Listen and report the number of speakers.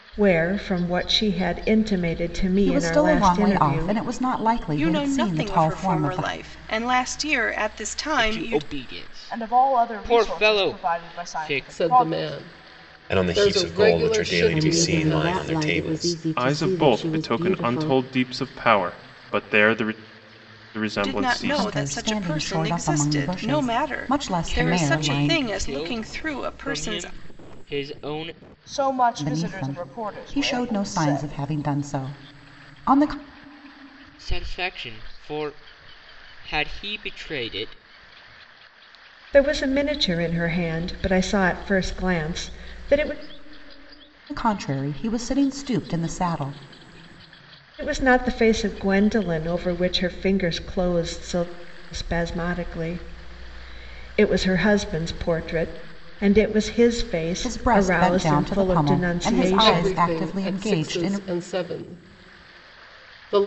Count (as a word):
nine